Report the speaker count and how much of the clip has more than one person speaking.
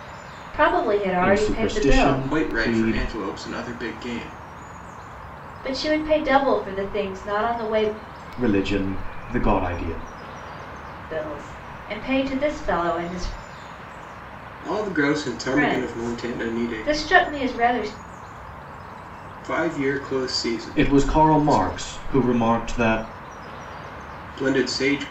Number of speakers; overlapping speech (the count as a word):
three, about 16%